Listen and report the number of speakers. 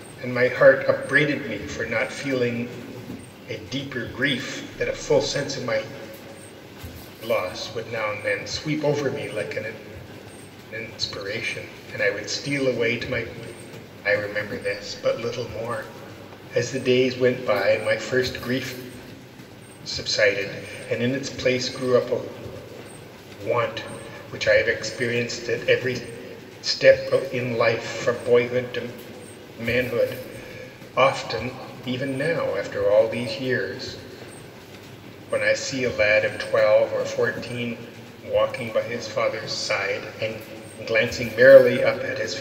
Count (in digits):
1